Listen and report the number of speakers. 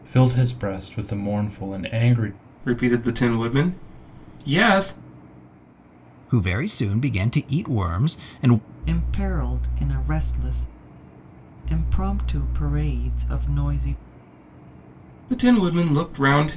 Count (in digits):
4